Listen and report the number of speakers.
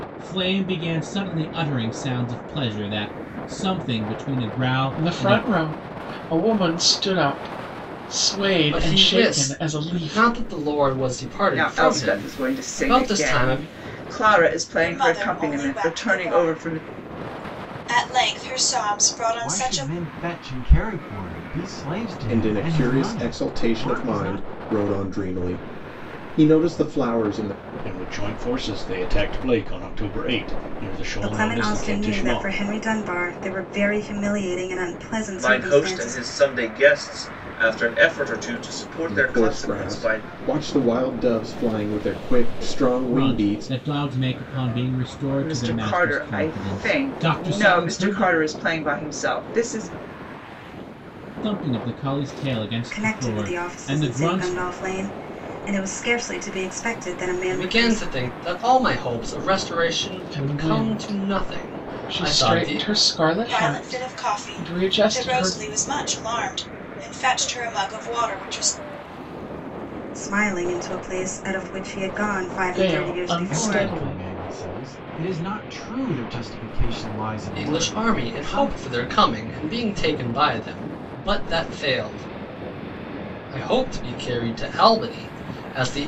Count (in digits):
10